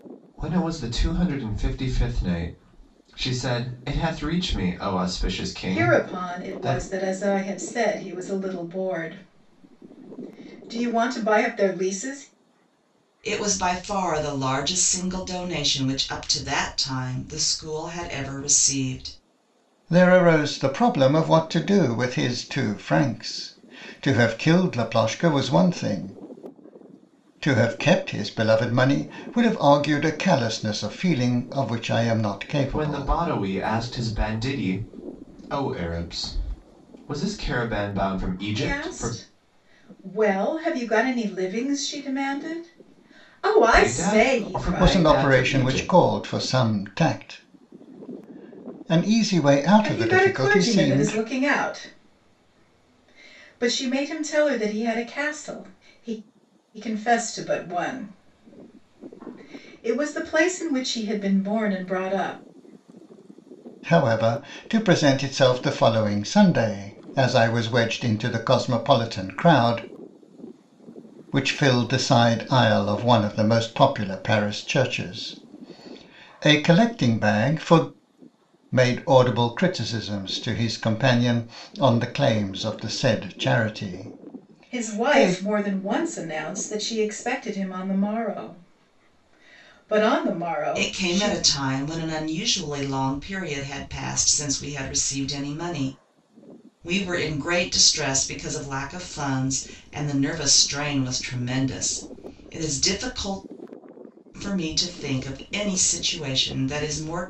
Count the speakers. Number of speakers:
4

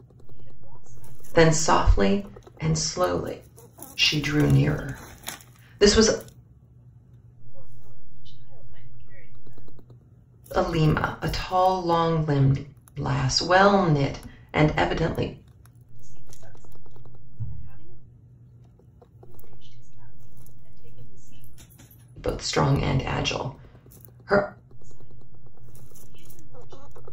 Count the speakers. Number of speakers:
2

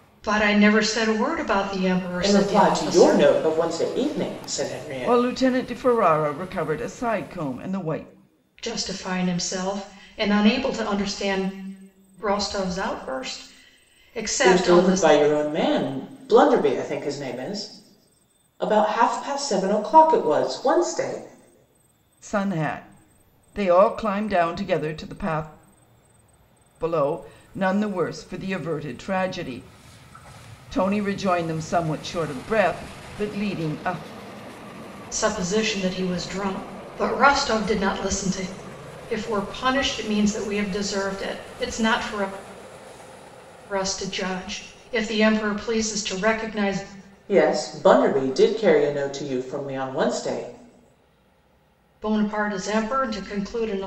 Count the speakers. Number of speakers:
3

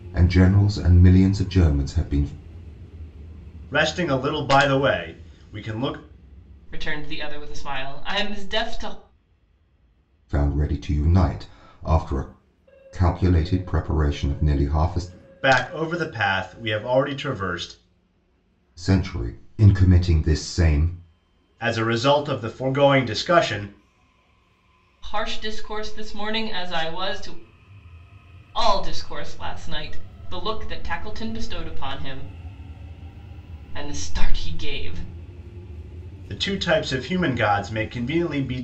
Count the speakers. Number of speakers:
3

